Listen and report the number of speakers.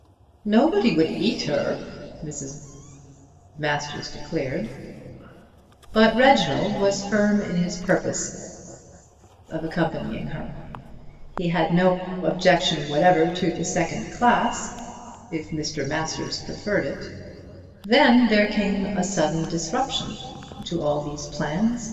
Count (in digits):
1